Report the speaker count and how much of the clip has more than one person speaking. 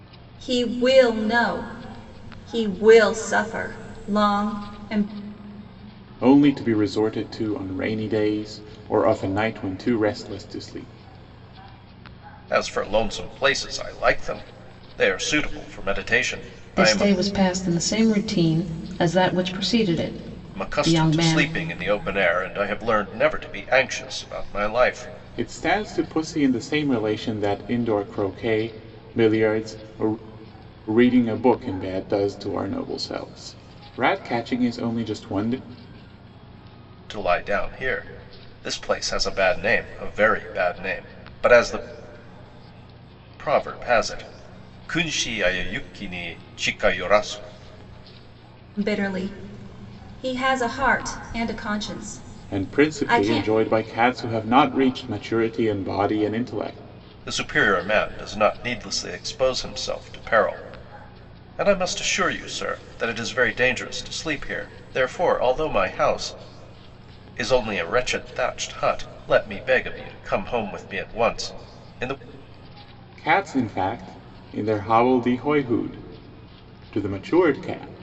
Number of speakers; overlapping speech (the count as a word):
four, about 3%